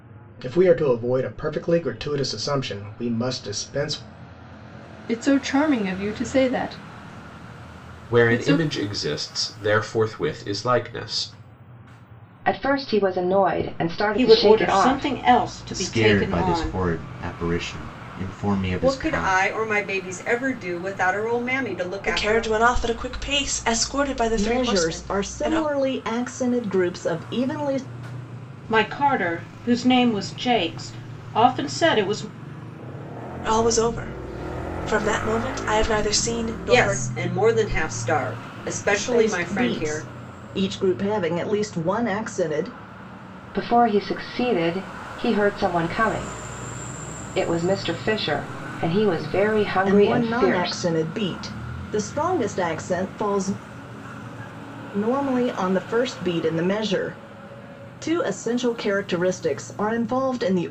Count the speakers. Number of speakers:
nine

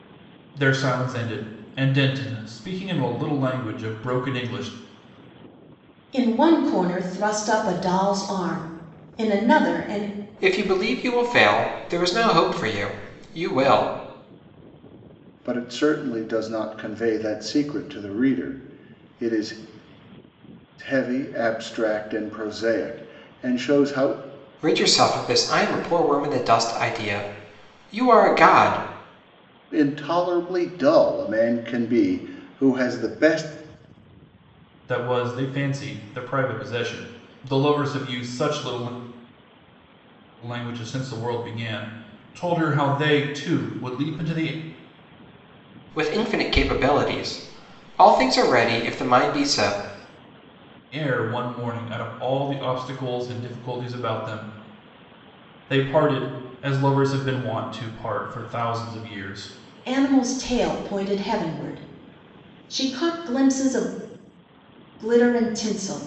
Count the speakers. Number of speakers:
four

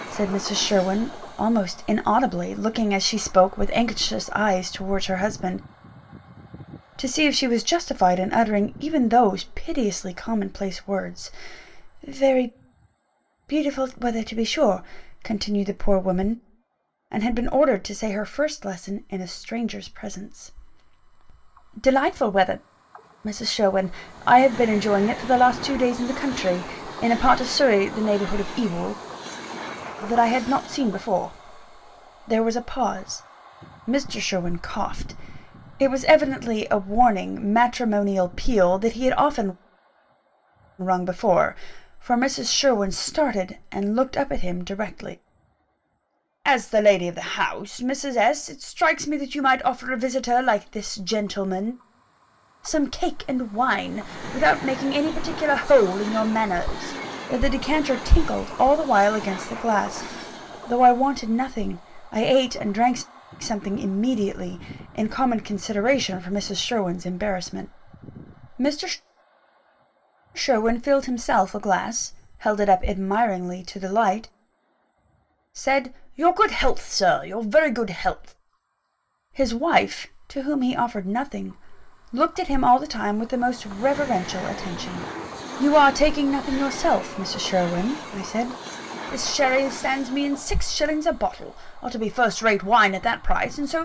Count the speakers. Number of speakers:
one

